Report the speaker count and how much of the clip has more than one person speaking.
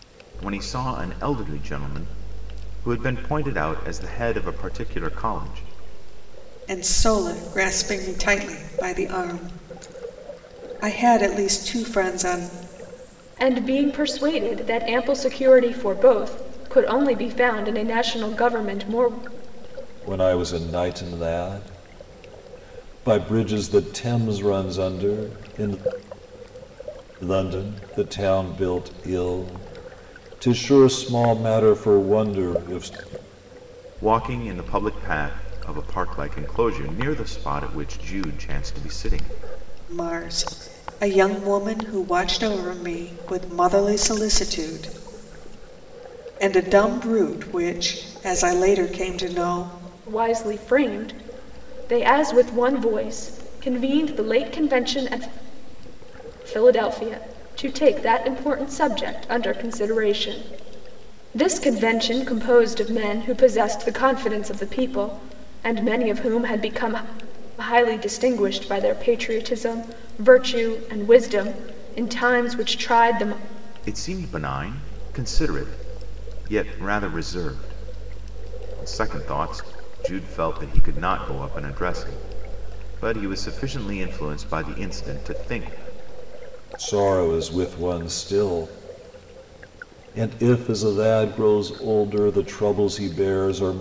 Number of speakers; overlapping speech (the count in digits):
4, no overlap